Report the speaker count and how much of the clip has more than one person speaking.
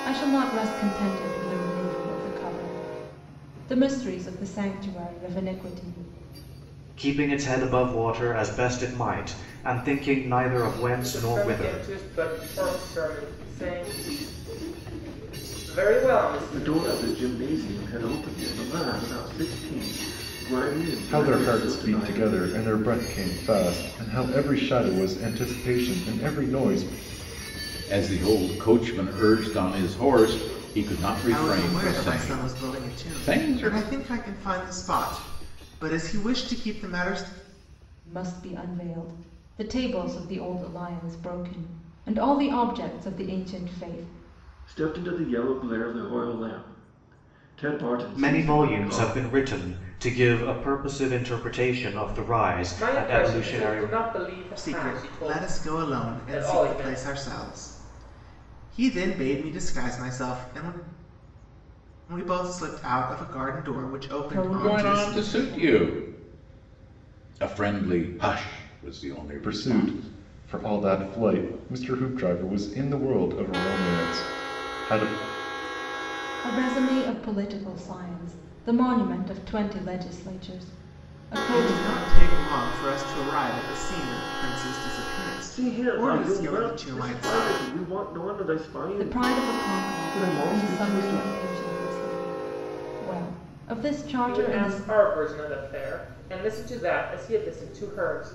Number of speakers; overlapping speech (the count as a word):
seven, about 19%